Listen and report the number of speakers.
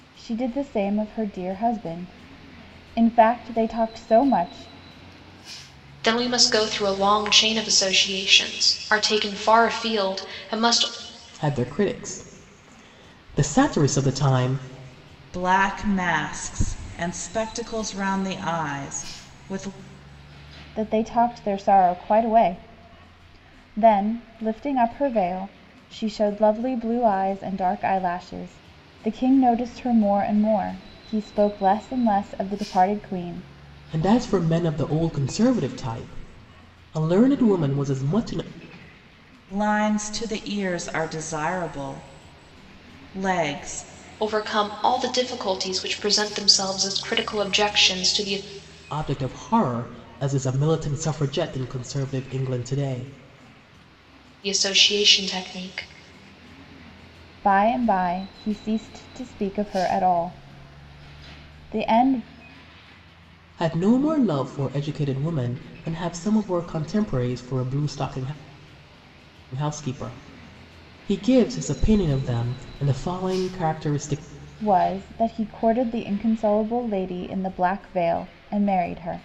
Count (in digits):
4